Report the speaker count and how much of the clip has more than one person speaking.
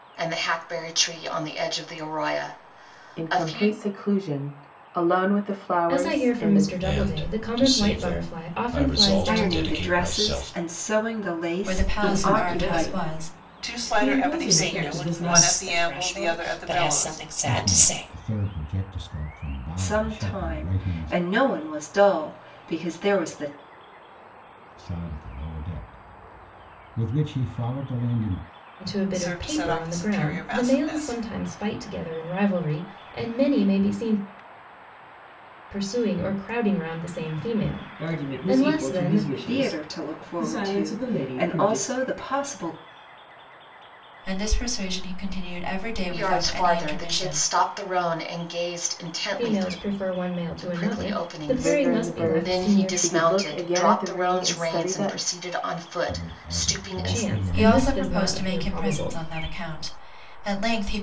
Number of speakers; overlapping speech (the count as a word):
ten, about 46%